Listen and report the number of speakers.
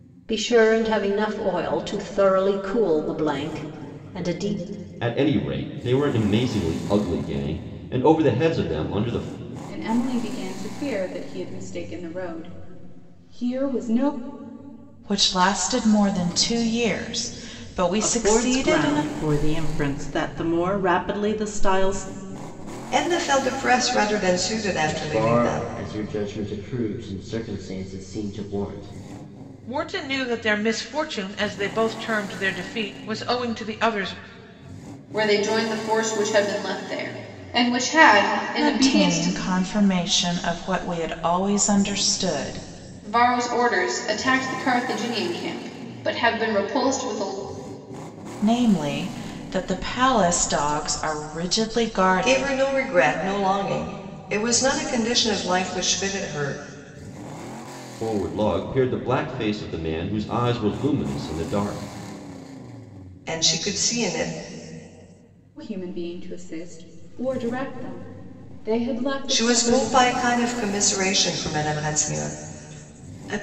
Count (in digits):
9